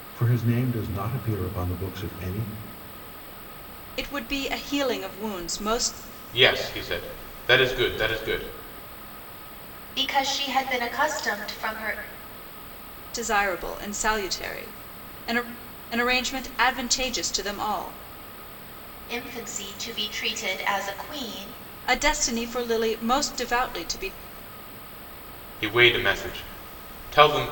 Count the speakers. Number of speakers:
4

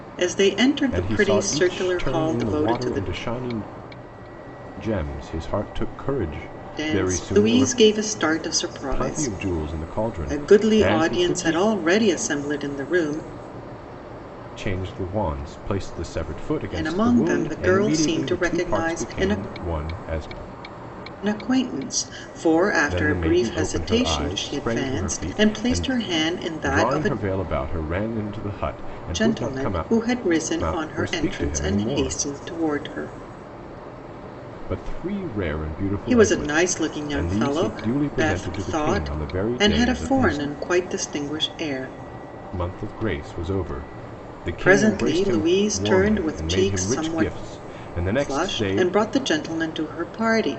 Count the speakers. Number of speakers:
2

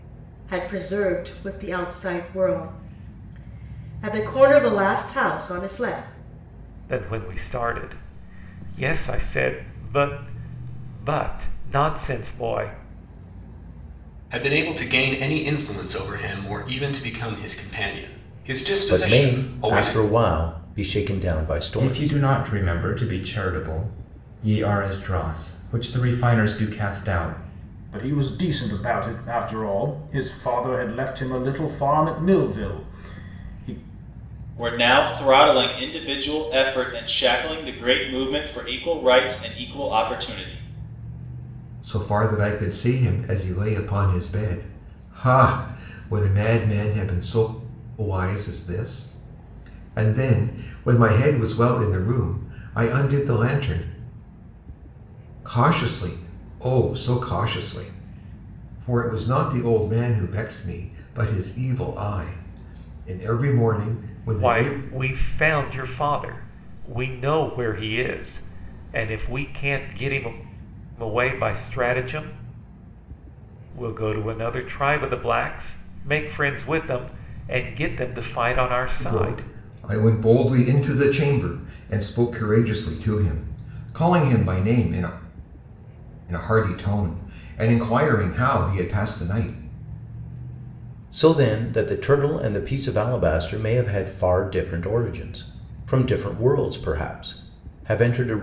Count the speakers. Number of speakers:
8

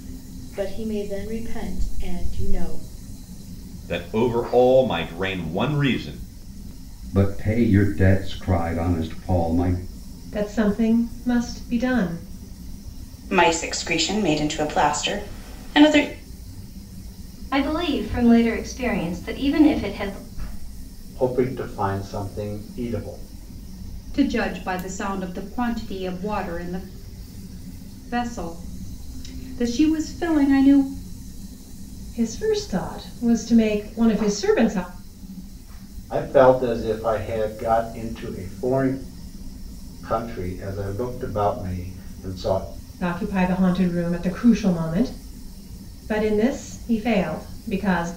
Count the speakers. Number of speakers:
8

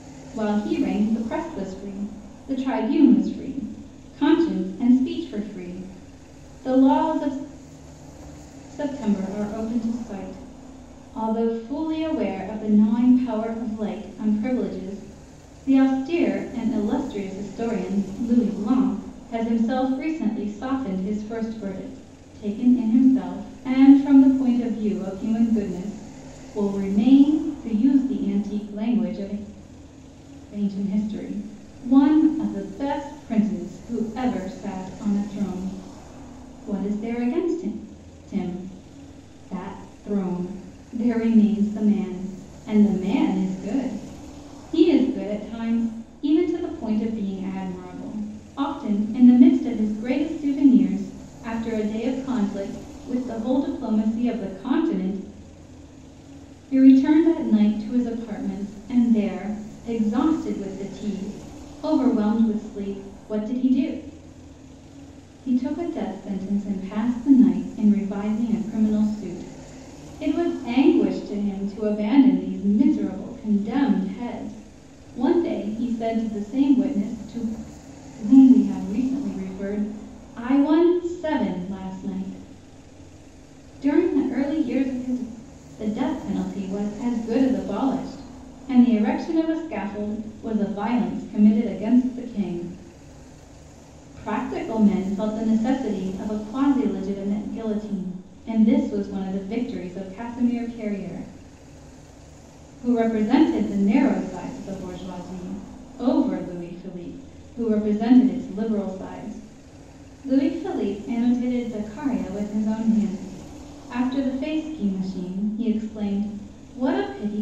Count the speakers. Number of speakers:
1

